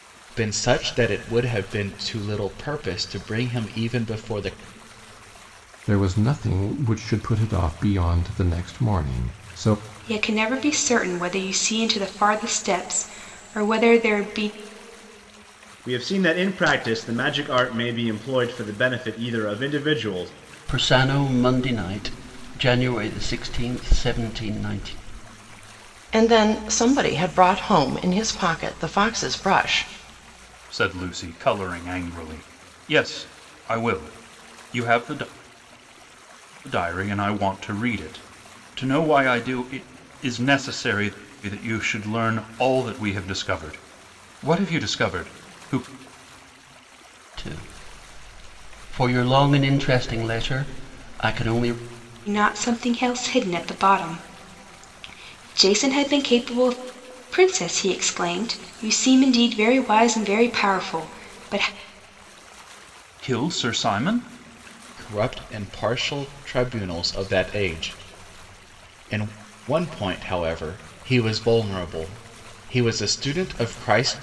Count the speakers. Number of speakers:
7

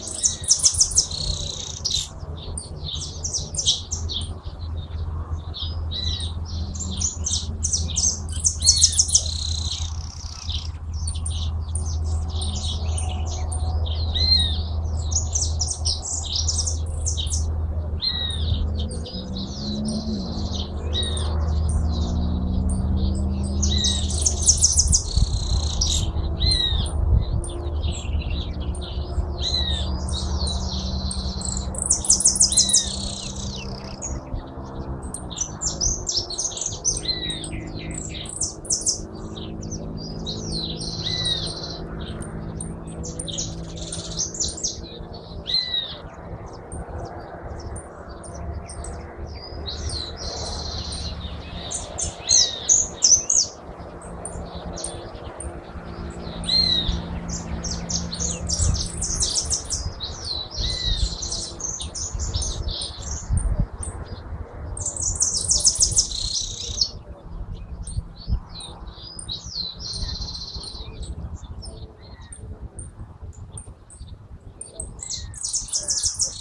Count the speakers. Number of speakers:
0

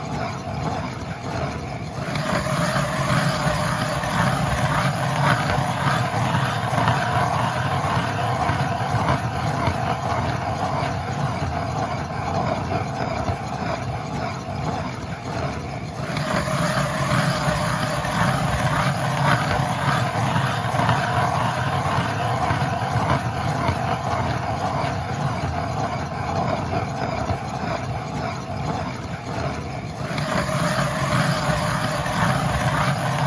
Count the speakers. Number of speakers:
0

